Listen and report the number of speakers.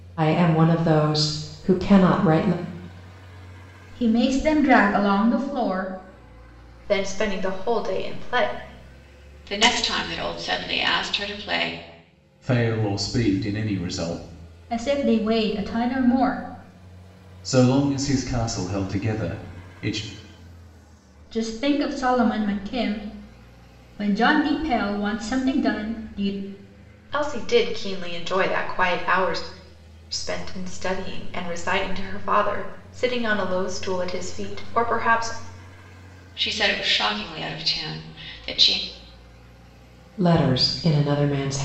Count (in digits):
5